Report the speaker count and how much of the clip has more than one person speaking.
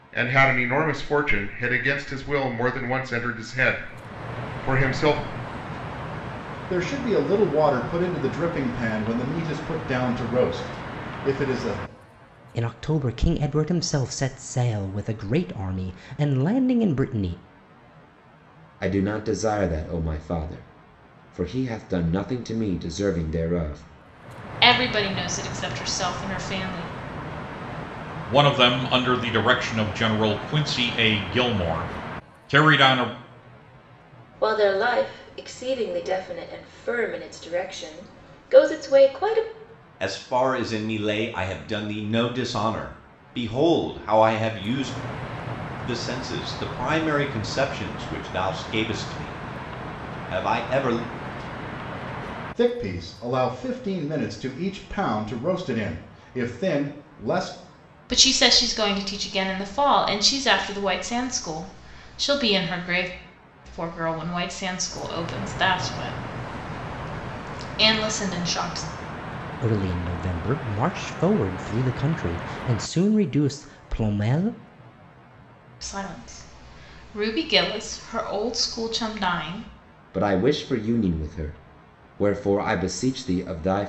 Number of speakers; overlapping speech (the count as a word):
eight, no overlap